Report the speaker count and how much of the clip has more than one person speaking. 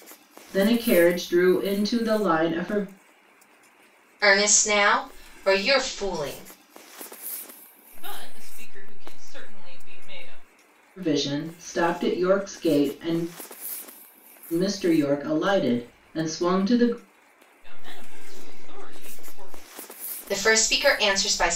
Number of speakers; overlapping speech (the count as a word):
three, no overlap